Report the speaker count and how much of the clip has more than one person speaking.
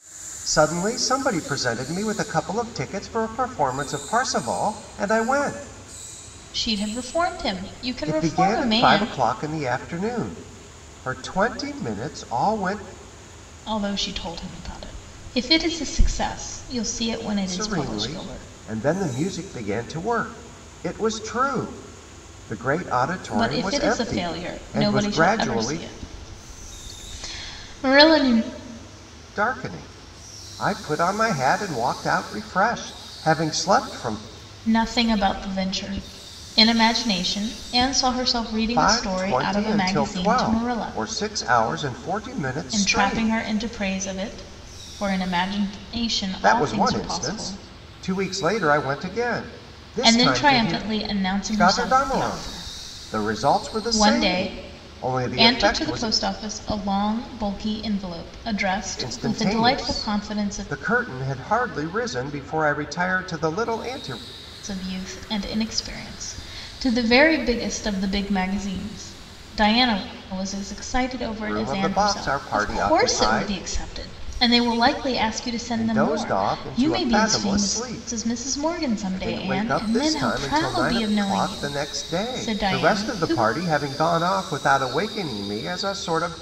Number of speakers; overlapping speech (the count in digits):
2, about 29%